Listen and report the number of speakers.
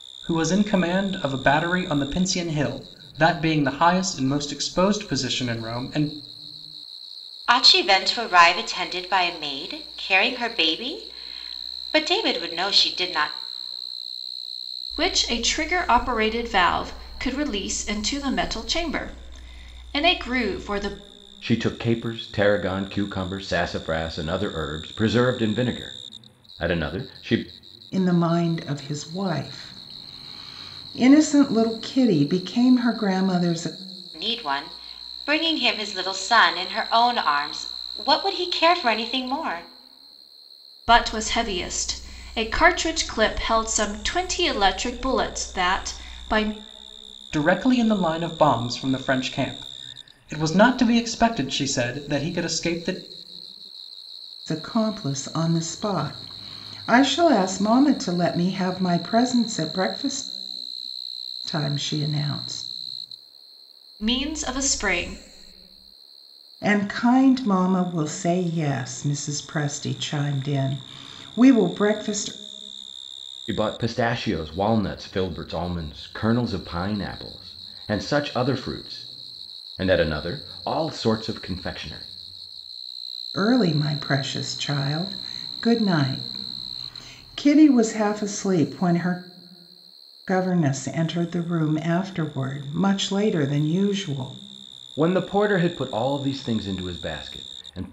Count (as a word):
five